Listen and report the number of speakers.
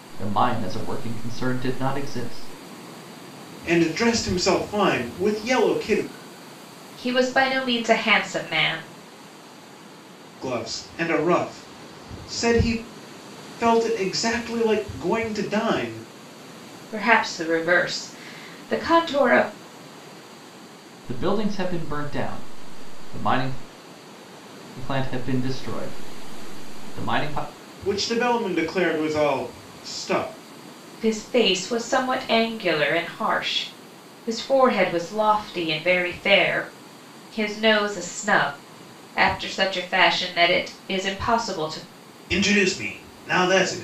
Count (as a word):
three